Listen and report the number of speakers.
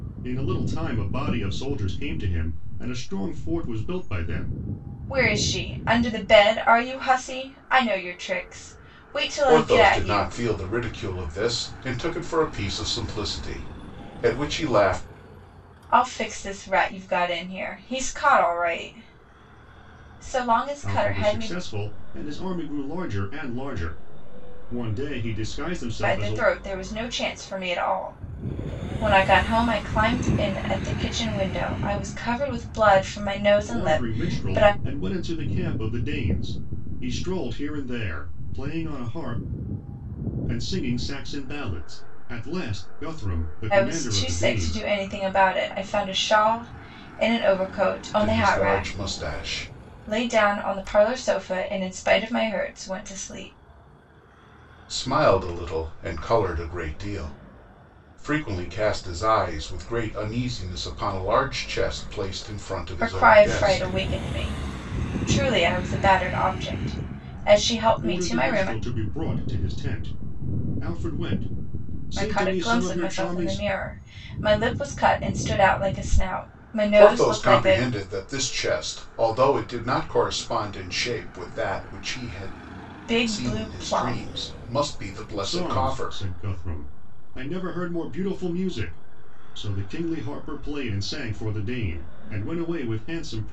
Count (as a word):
three